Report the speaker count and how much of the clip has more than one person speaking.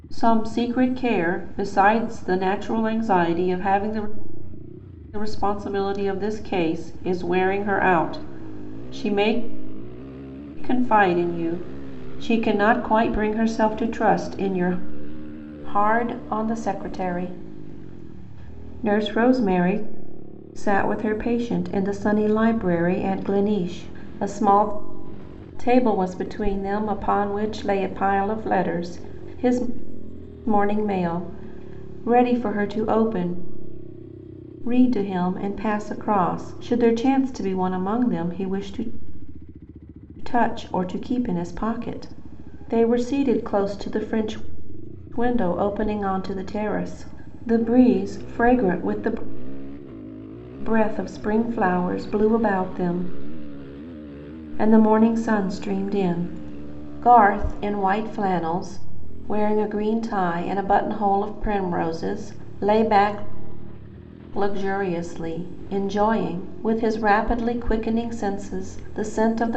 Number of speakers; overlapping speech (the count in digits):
1, no overlap